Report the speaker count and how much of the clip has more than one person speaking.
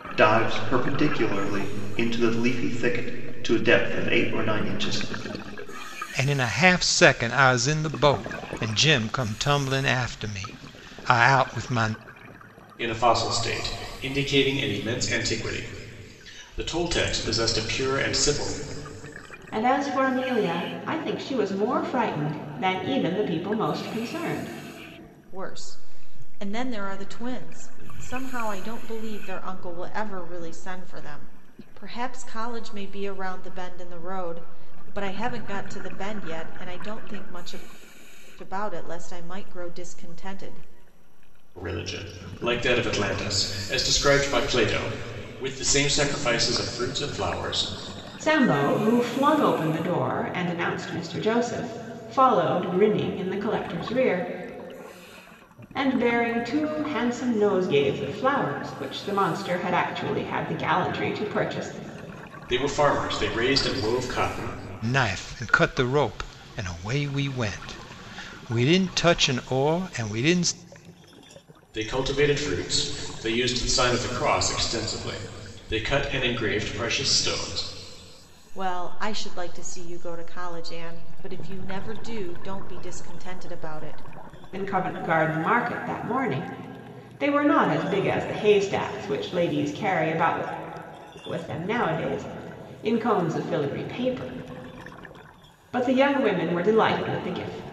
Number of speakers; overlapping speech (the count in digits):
5, no overlap